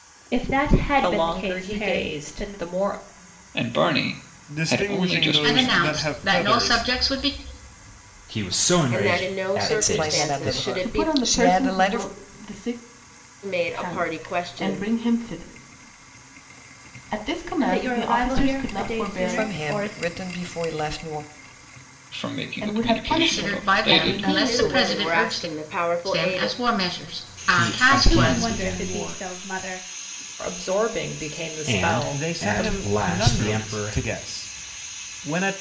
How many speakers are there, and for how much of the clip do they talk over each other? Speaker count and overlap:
9, about 52%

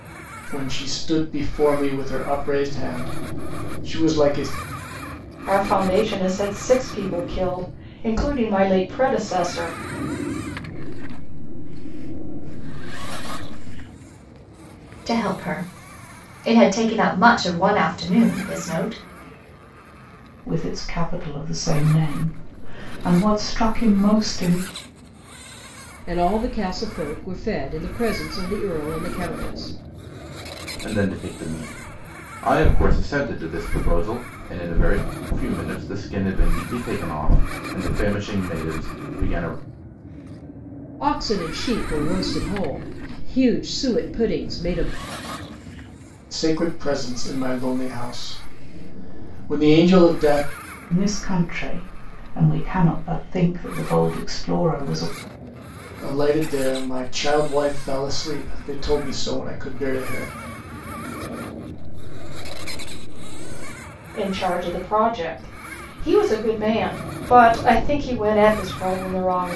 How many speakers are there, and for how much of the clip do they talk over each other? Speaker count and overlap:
7, no overlap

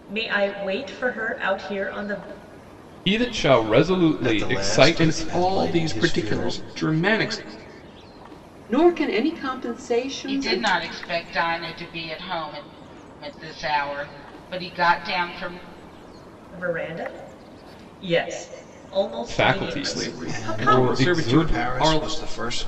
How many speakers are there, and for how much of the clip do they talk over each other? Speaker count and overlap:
6, about 25%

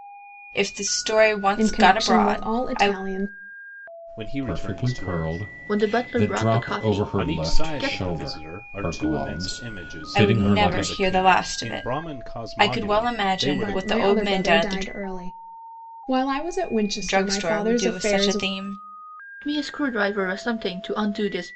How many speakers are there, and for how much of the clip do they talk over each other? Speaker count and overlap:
5, about 57%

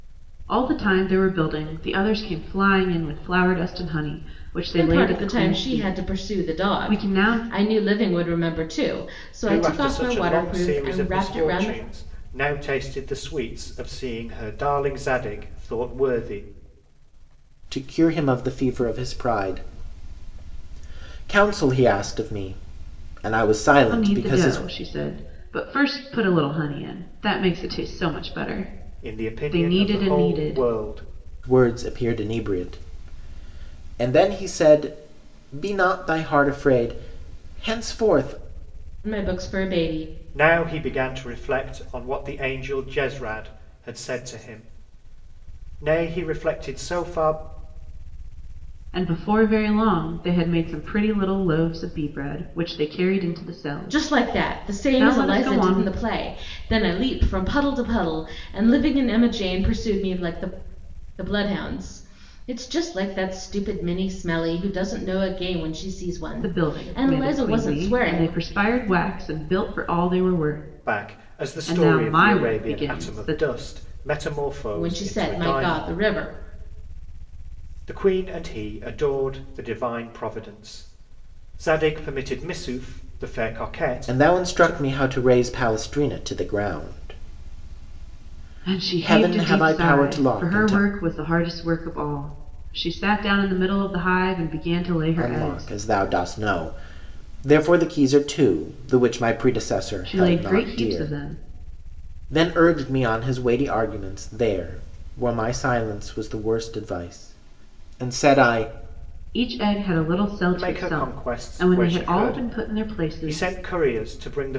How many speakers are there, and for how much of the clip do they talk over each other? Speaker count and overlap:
4, about 20%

